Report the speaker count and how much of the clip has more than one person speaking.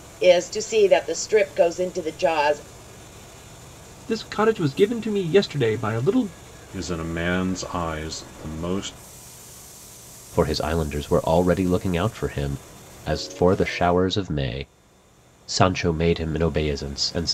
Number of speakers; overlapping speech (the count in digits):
4, no overlap